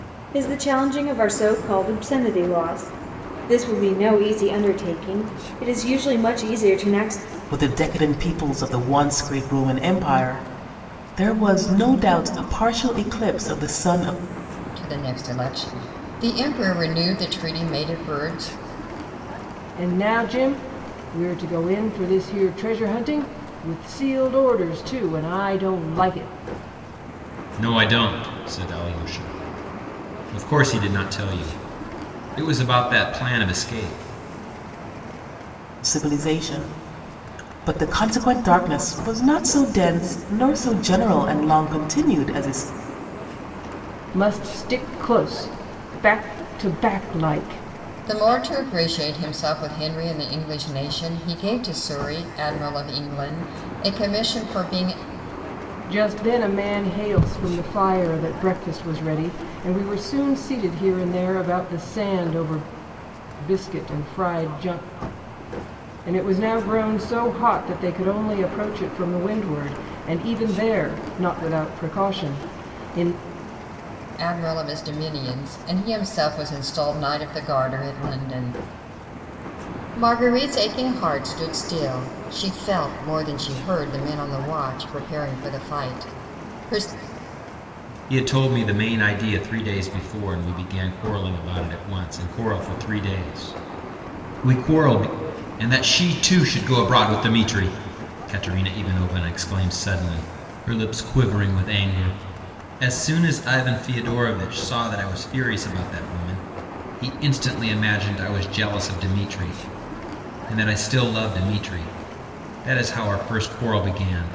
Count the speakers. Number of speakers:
five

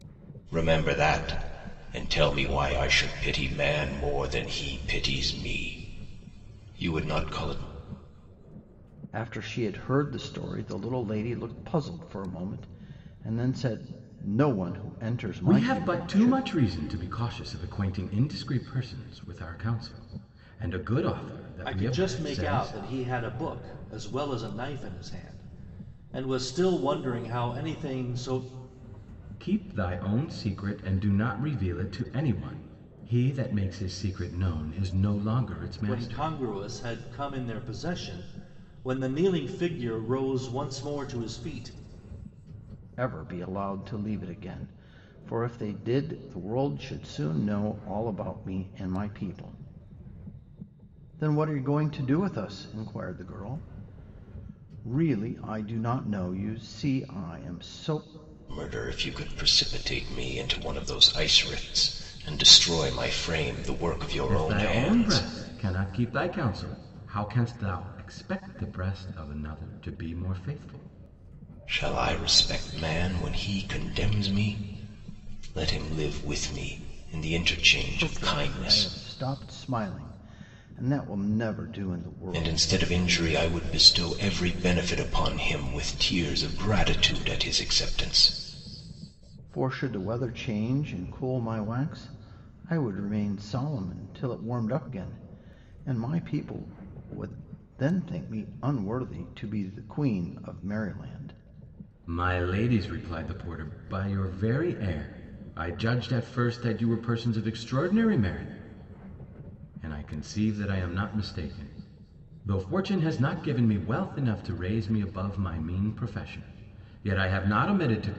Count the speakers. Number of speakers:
four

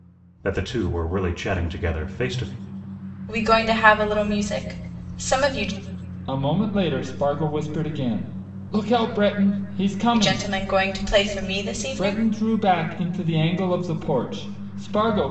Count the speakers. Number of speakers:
three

